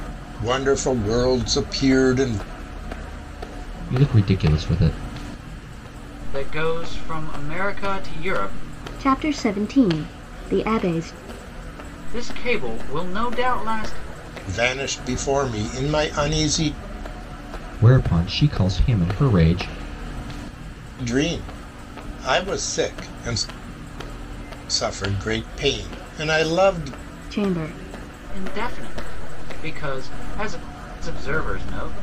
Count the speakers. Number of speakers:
4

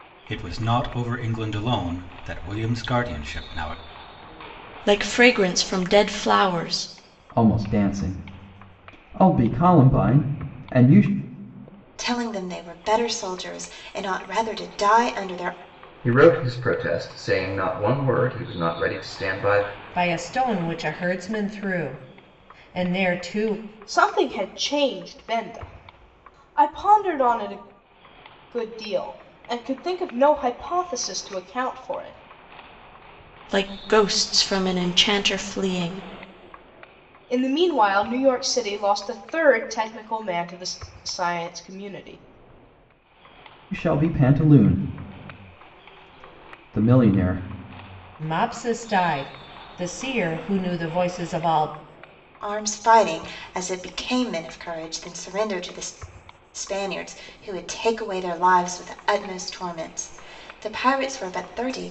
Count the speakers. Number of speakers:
7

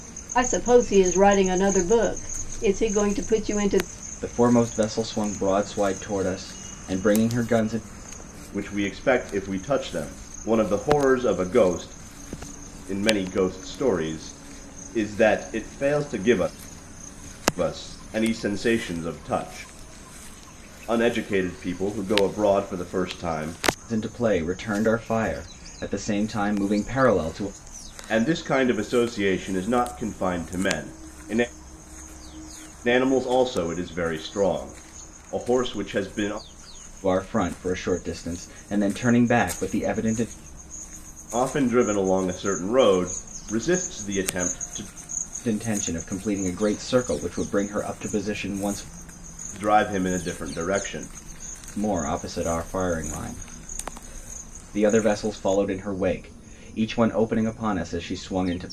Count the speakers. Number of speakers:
3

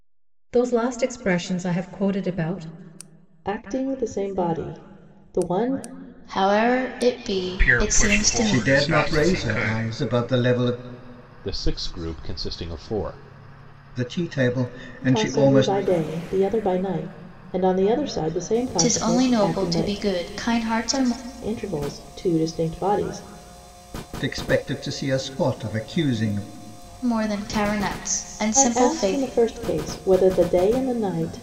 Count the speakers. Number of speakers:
6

